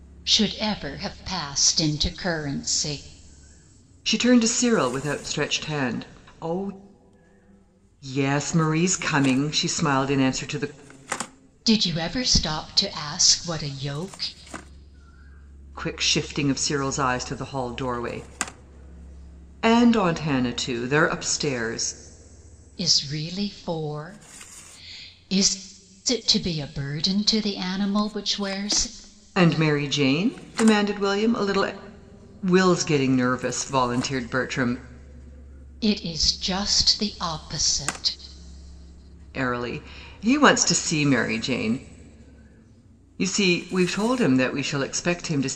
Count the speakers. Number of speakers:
two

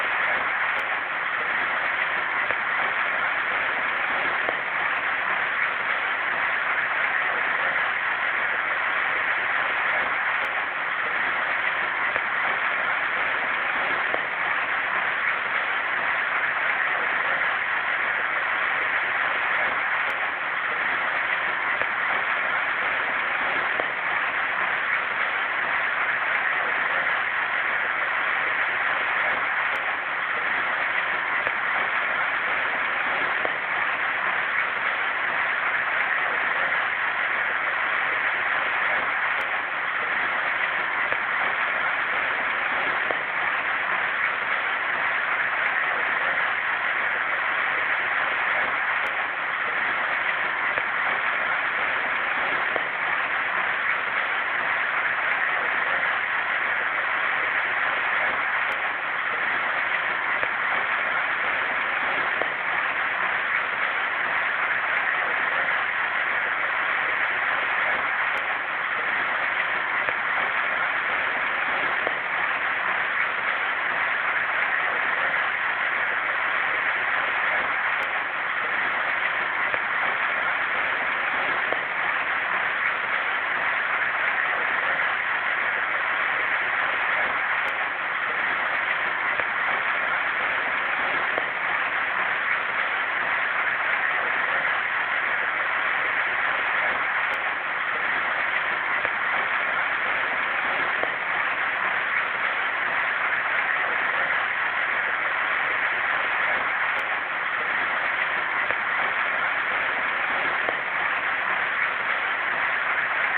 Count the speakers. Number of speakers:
zero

